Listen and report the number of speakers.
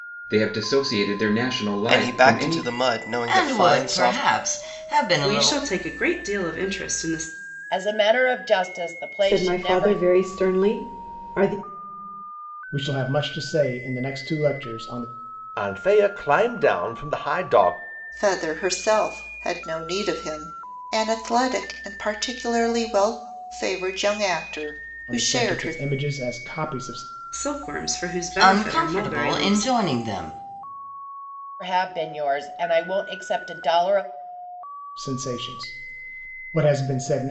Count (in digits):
9